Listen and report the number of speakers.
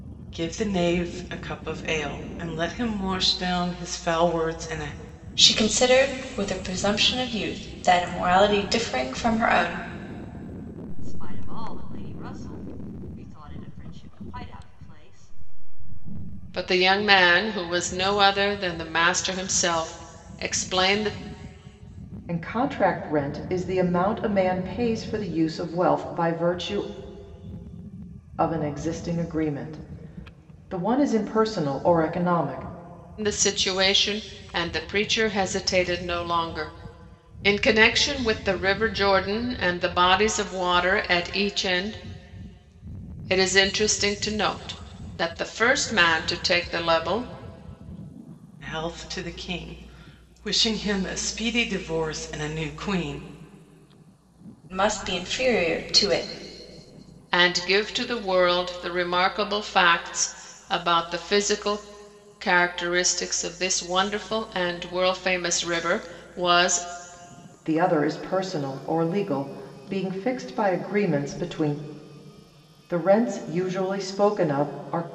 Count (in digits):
5